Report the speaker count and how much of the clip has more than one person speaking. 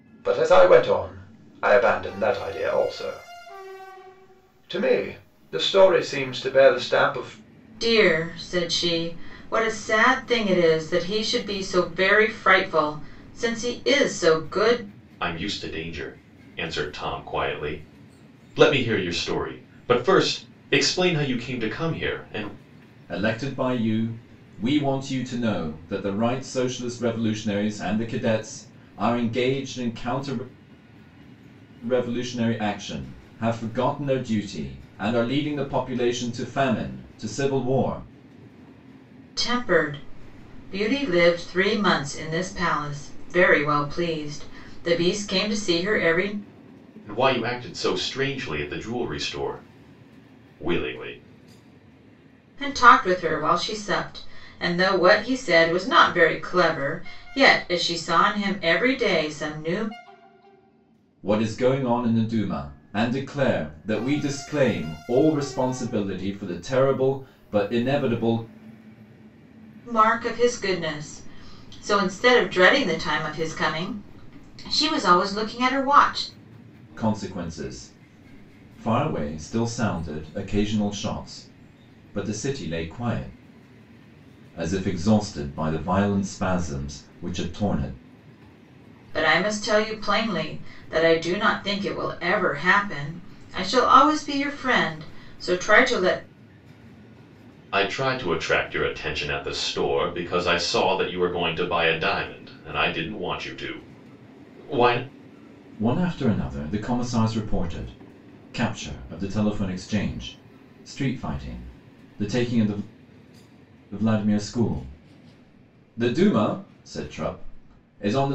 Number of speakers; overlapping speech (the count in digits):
4, no overlap